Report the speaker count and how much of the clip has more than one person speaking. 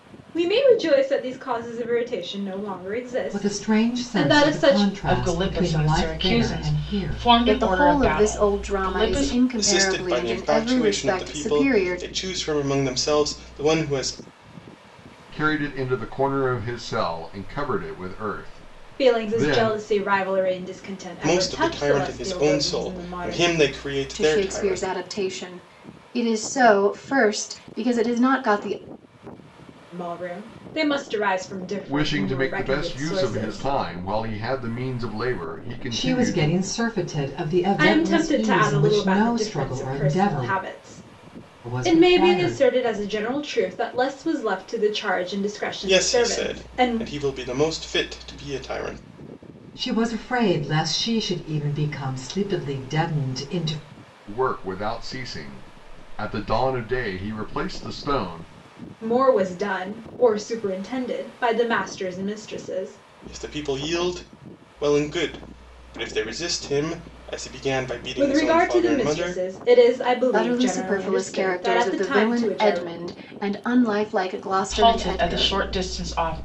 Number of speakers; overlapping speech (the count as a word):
six, about 32%